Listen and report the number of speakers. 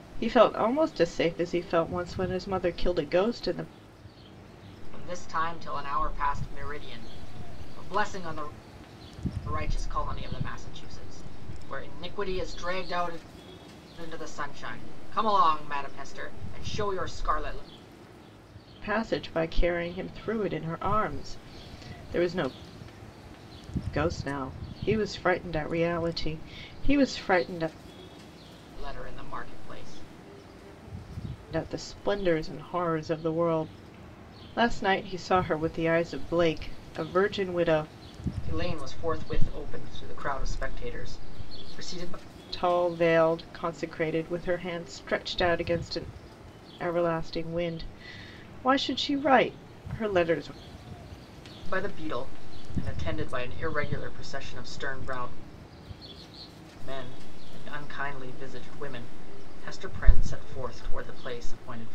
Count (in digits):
2